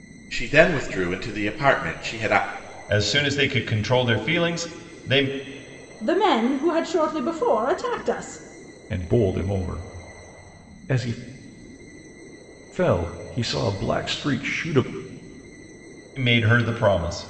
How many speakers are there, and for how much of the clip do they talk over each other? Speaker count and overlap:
four, no overlap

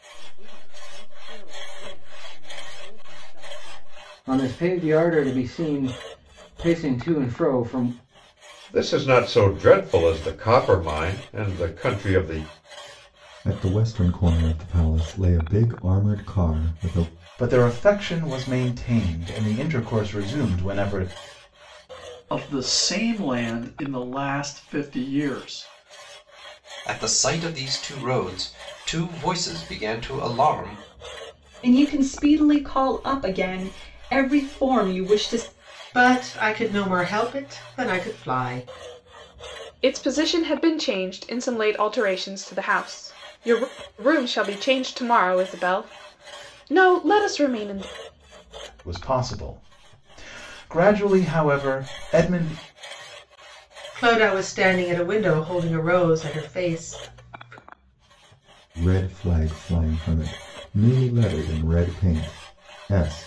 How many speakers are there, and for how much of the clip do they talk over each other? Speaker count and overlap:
ten, no overlap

